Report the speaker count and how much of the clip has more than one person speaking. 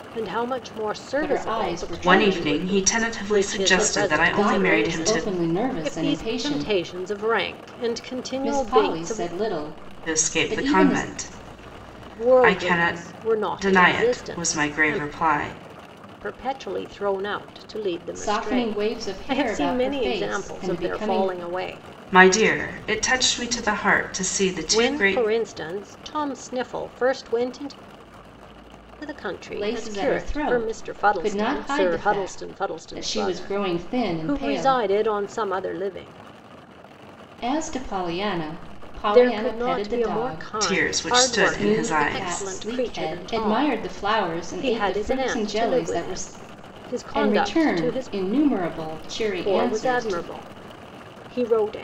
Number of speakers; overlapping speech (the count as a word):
three, about 53%